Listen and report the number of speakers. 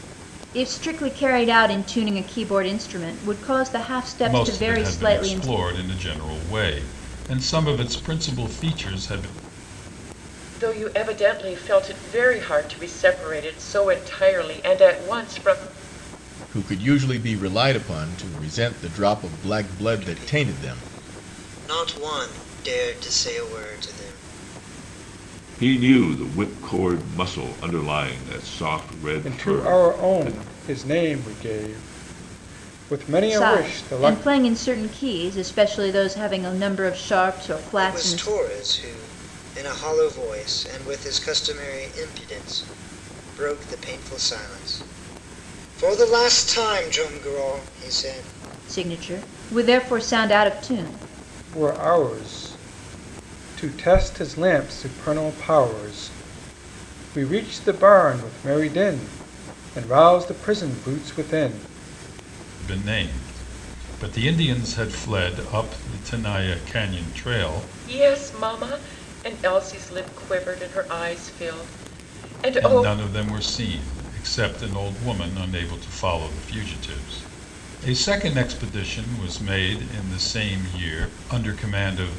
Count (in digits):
7